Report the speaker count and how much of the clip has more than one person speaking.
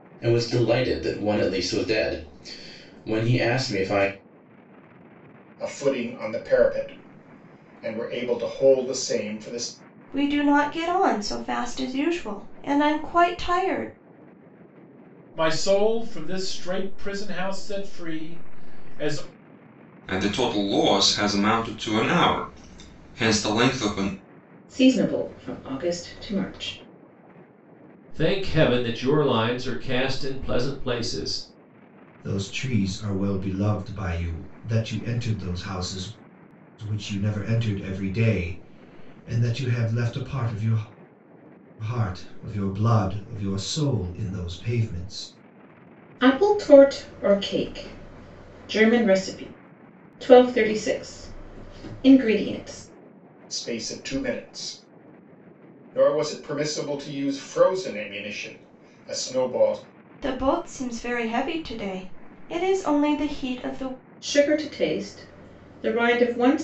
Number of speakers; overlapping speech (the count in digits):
8, no overlap